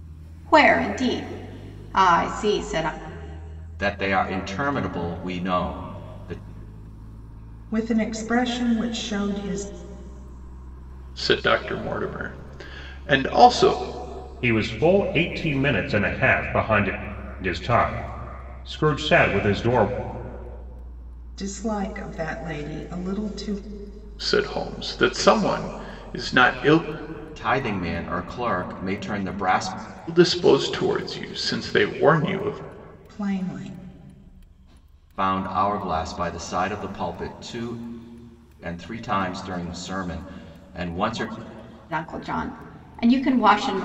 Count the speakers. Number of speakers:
5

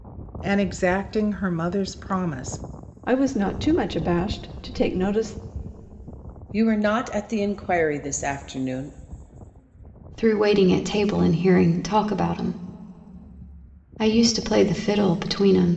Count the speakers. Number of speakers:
4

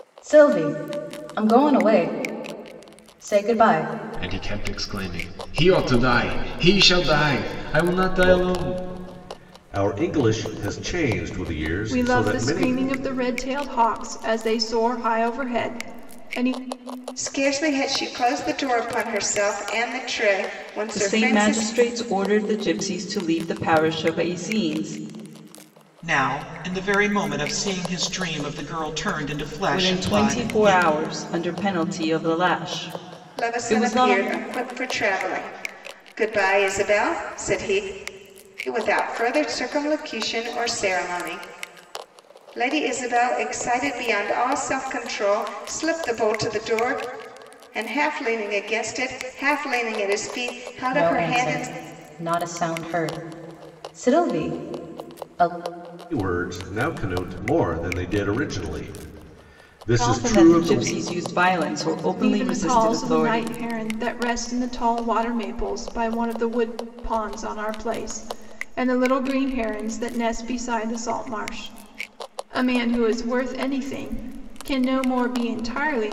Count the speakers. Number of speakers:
7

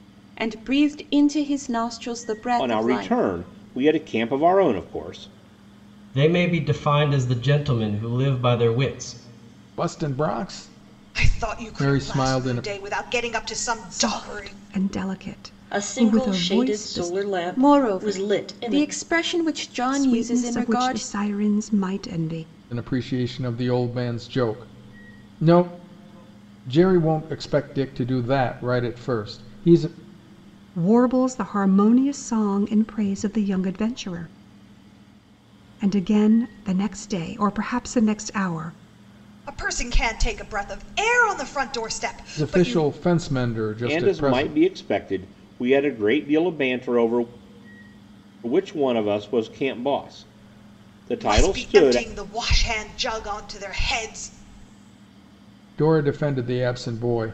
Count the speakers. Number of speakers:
7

